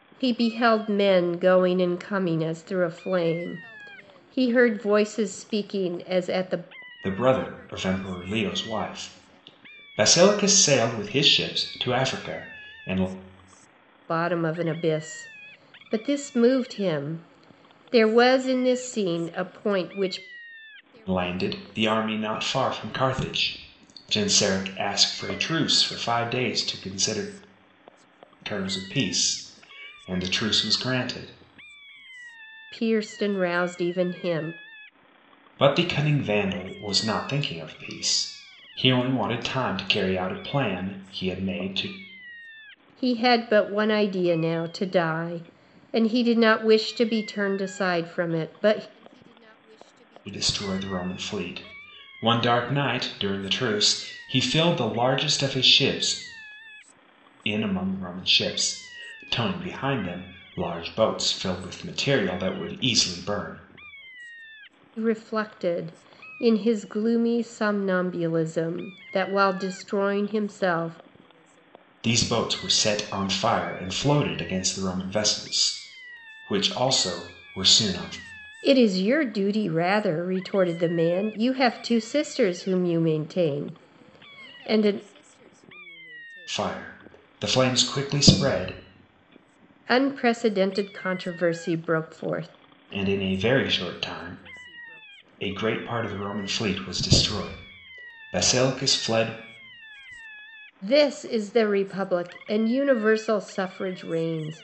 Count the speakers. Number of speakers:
2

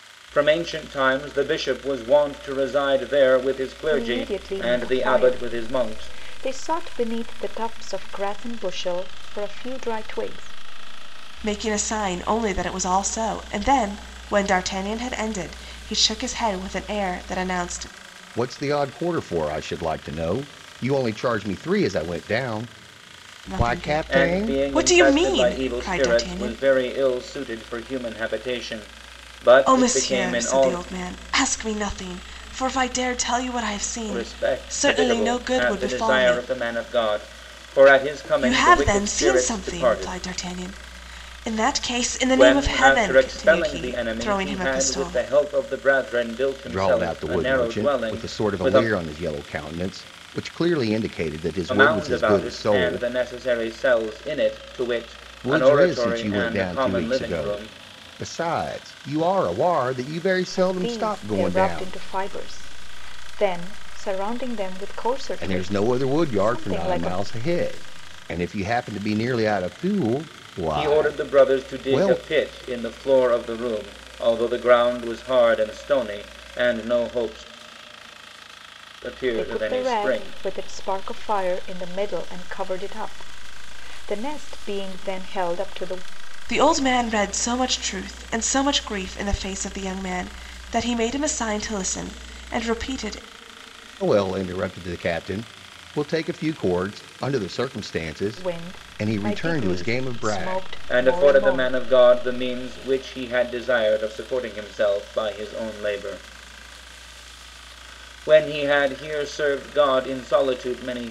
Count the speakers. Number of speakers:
4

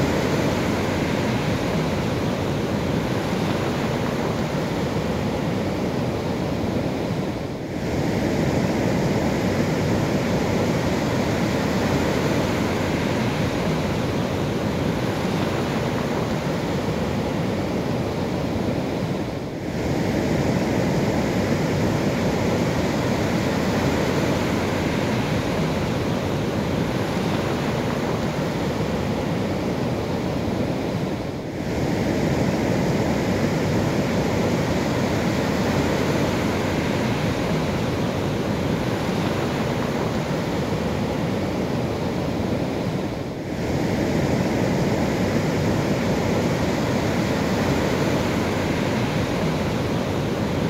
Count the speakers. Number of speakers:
0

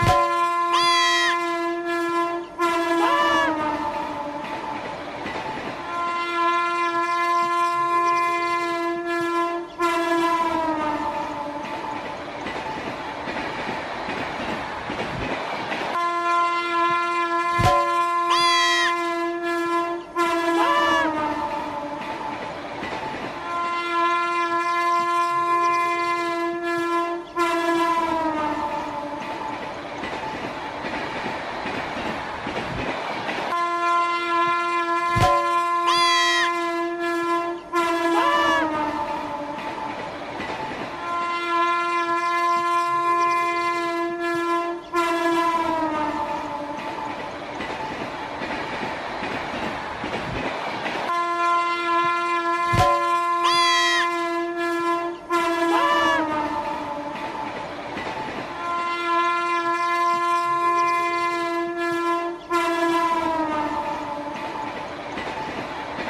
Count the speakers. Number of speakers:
0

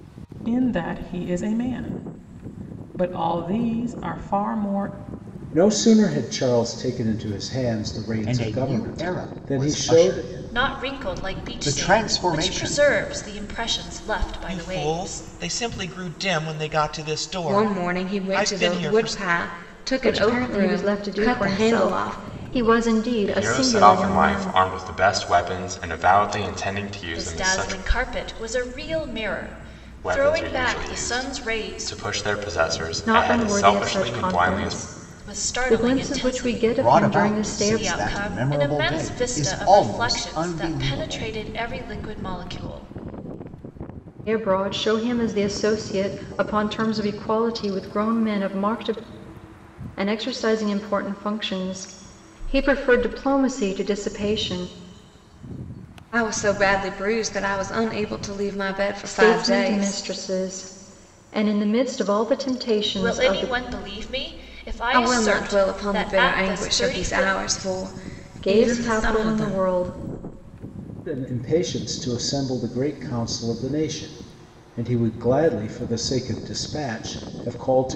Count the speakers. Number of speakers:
8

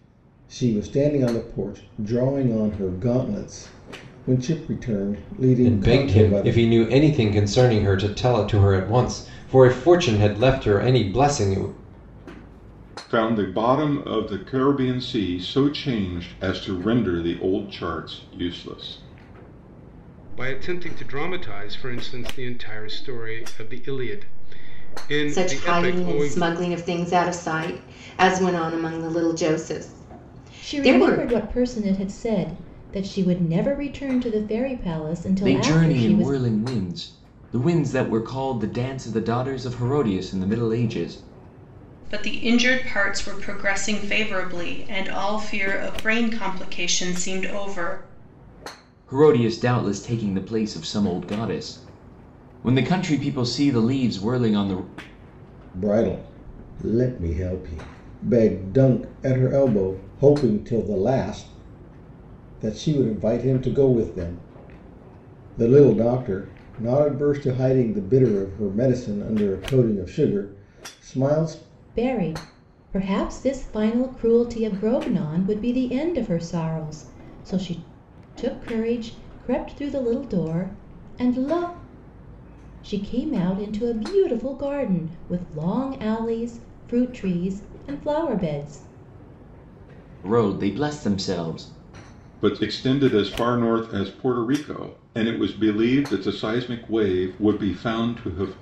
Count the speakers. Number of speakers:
8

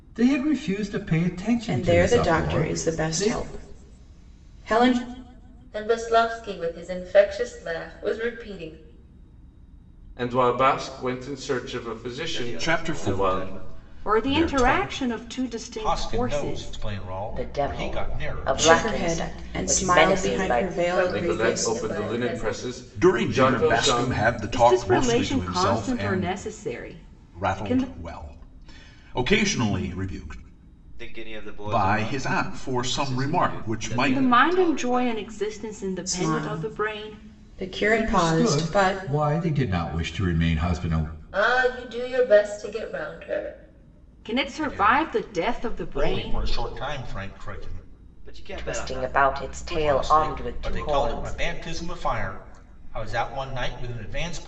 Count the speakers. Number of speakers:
9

